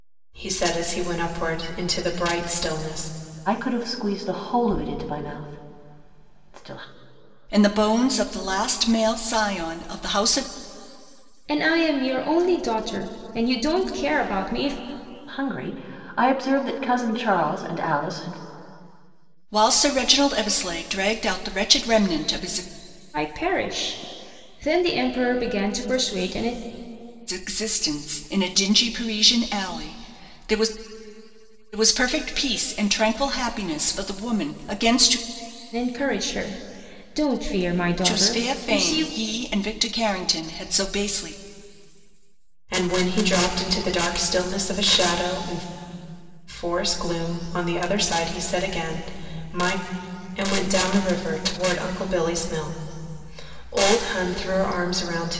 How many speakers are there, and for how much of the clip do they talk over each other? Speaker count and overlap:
four, about 2%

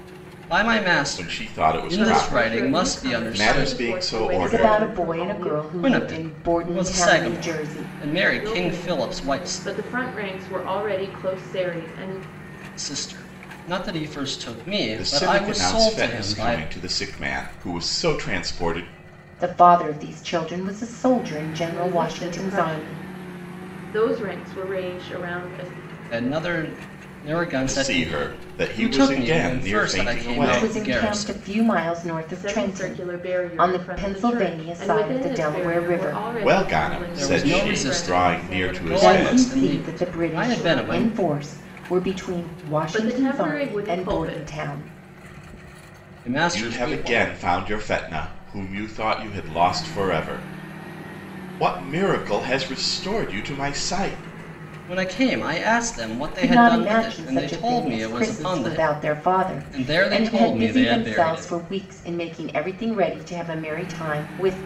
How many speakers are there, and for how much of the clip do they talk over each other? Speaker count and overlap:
four, about 49%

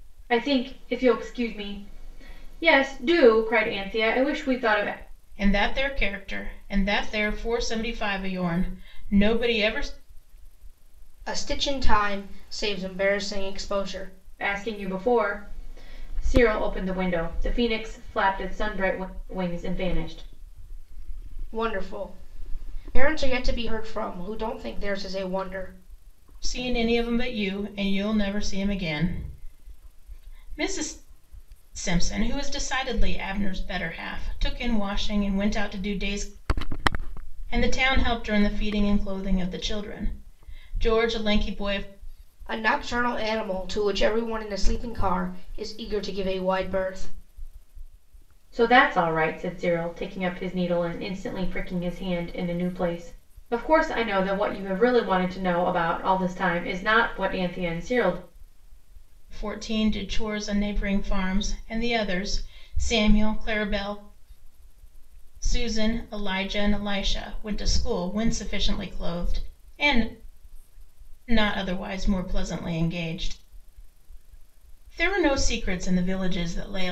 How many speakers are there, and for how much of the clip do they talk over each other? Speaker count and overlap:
three, no overlap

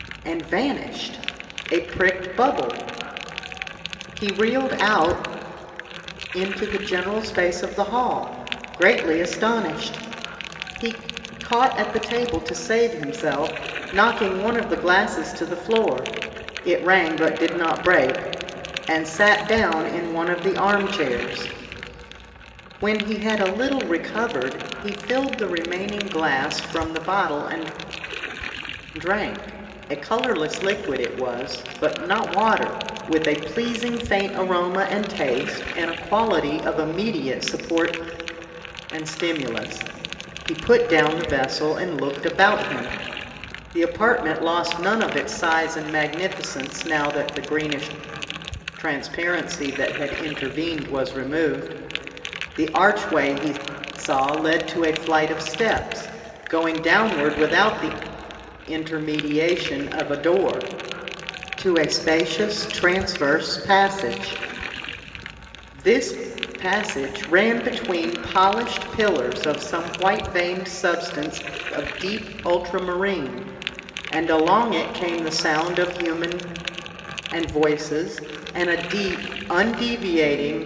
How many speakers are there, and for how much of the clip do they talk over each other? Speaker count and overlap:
one, no overlap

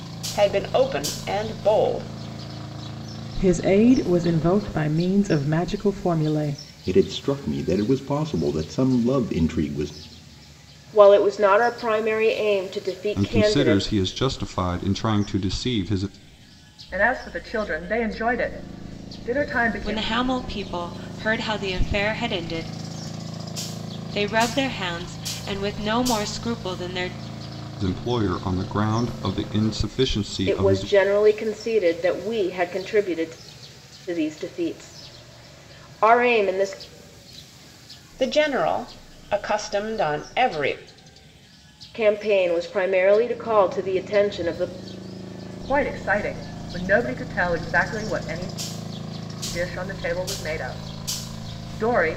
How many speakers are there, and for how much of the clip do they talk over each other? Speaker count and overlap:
seven, about 3%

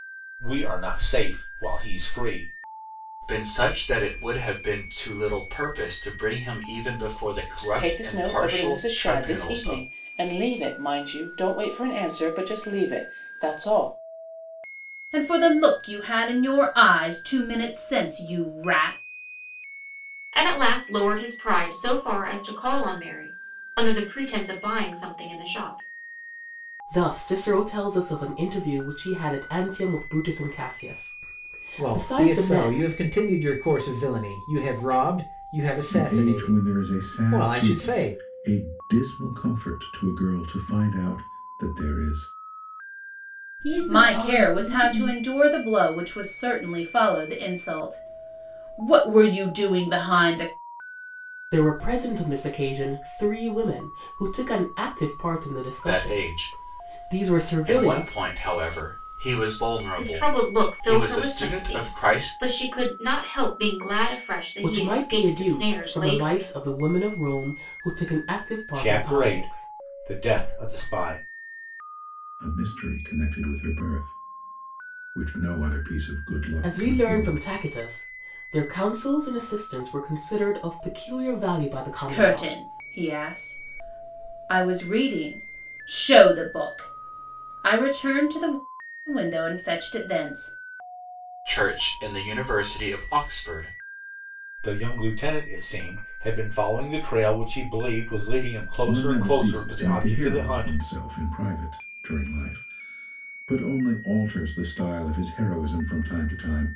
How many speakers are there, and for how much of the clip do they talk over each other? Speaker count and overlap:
nine, about 17%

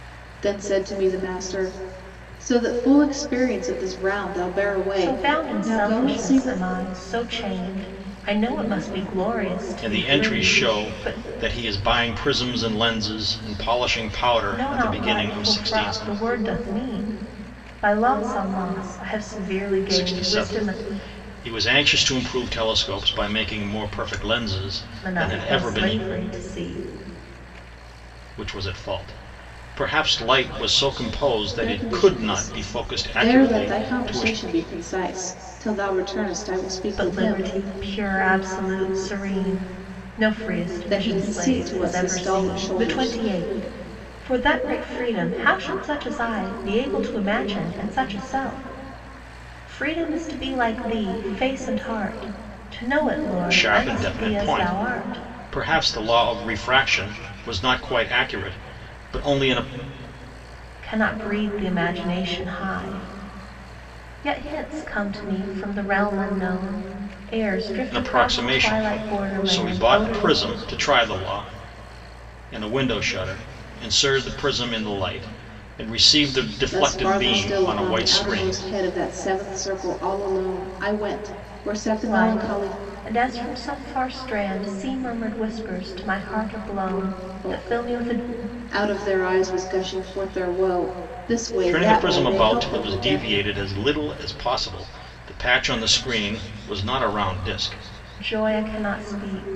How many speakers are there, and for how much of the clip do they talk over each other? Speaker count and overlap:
three, about 23%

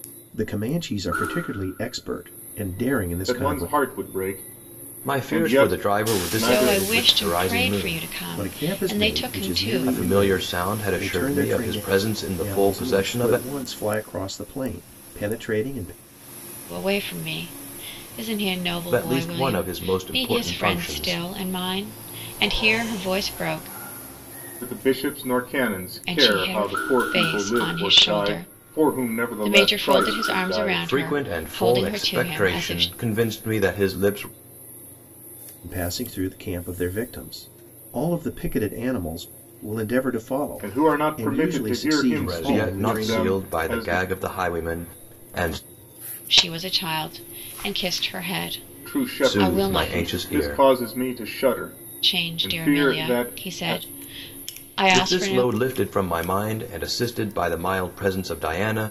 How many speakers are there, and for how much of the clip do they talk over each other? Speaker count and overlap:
four, about 41%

